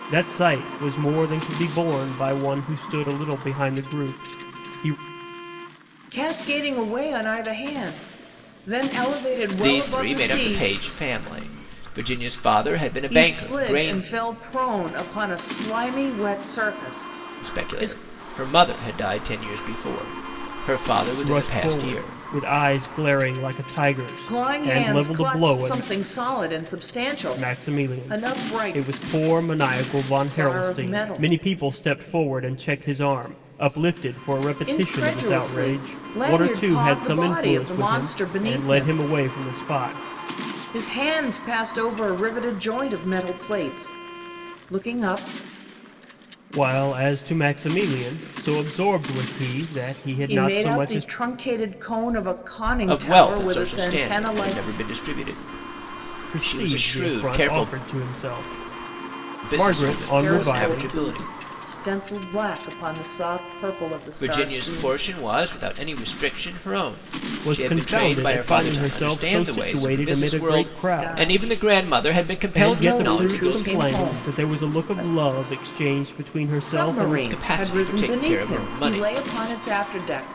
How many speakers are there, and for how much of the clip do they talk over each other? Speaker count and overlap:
3, about 36%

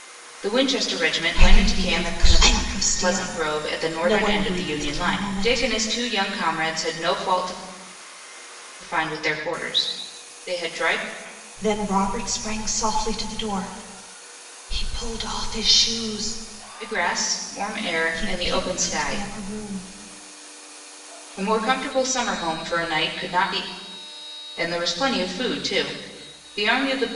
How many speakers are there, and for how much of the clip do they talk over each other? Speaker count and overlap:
2, about 16%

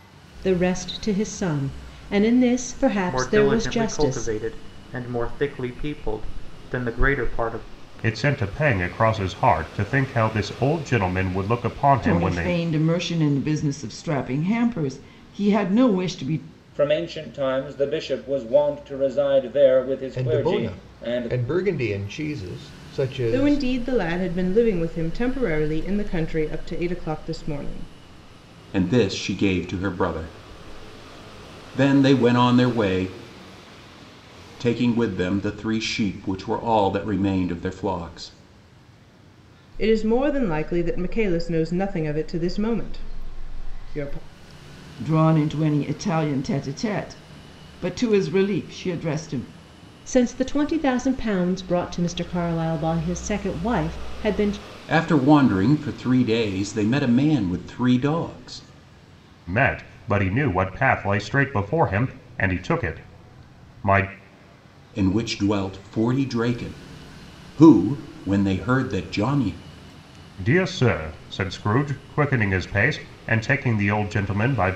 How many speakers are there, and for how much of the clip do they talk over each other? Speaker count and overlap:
8, about 5%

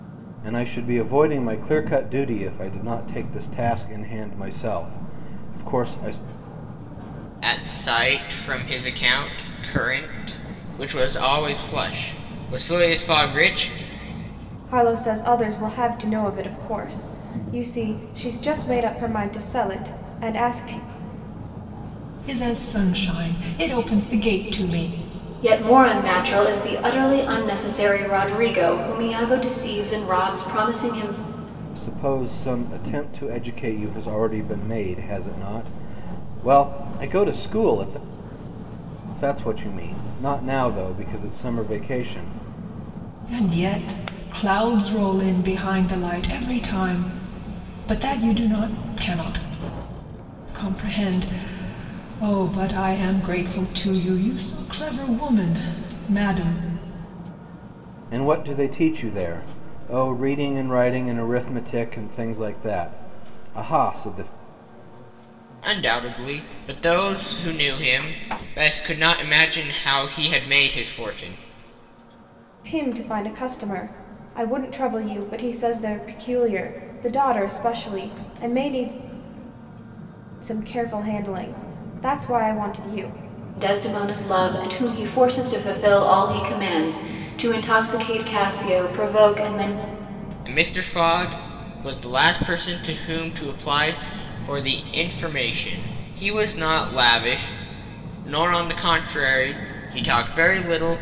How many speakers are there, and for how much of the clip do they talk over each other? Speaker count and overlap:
5, no overlap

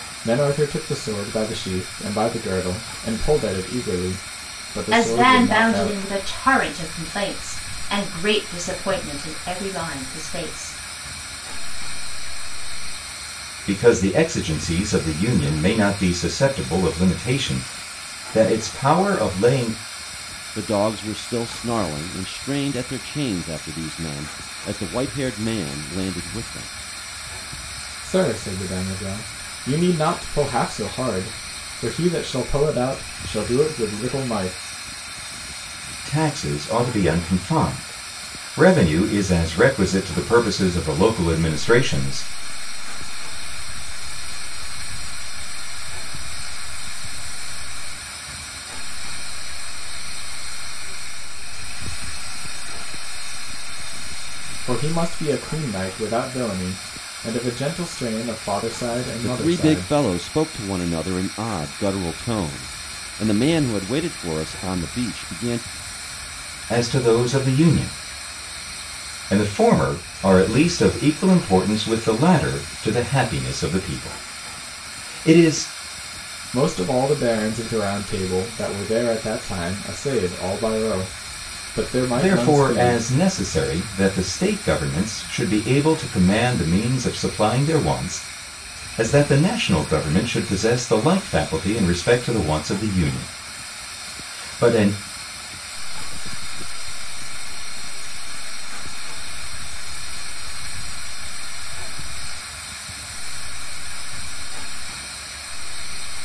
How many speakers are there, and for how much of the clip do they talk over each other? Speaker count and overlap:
5, about 4%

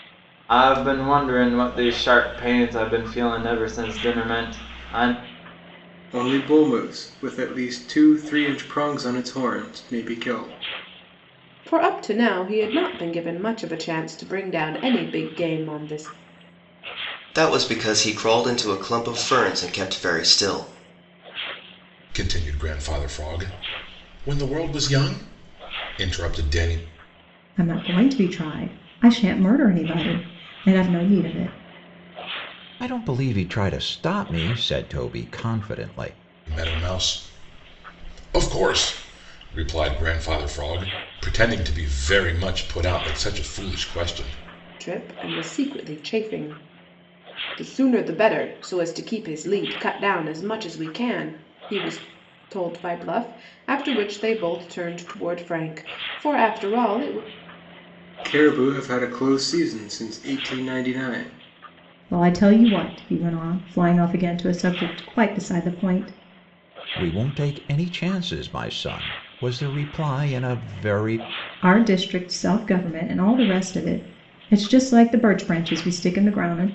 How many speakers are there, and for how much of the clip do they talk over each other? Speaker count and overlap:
7, no overlap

